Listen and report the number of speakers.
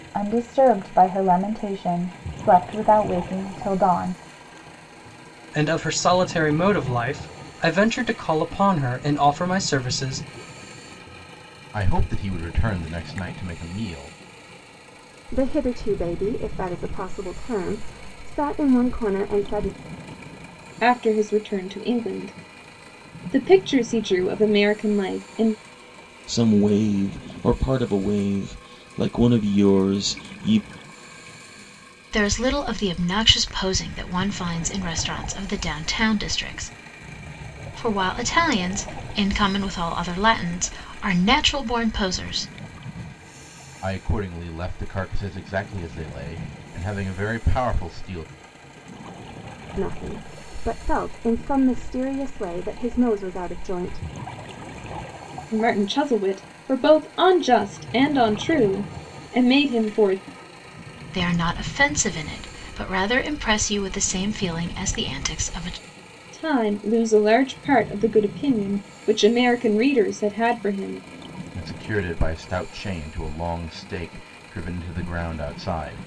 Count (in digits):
7